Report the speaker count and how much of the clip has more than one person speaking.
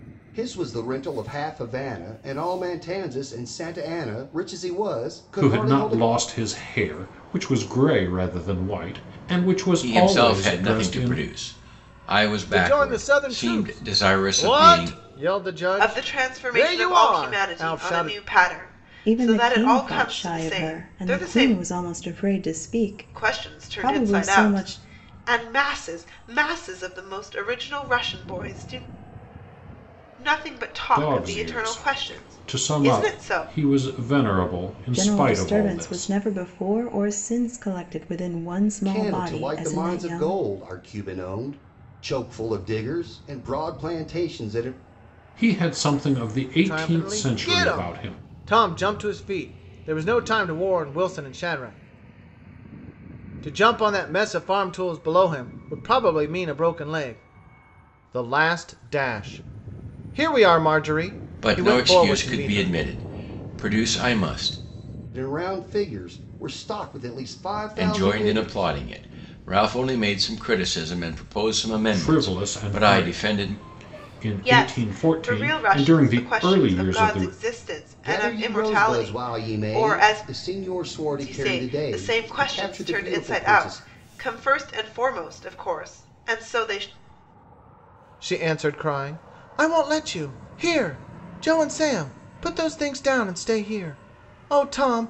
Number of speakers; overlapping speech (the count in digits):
6, about 32%